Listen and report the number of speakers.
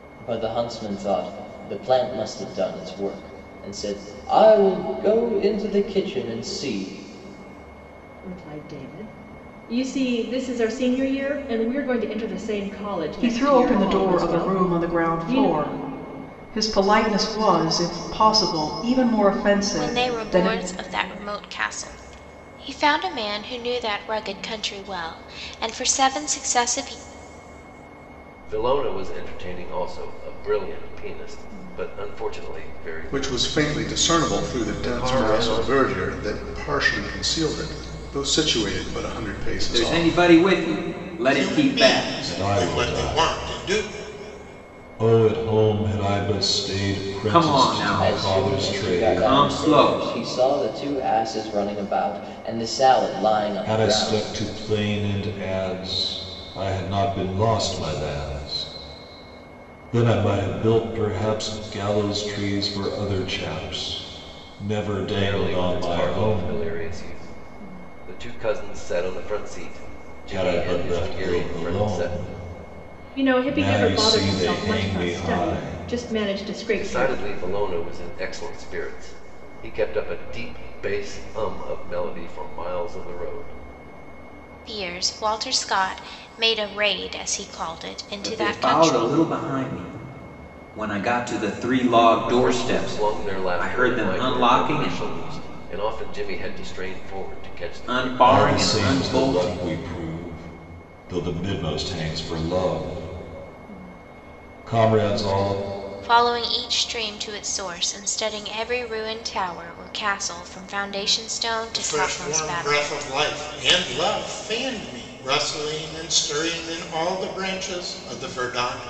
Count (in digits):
9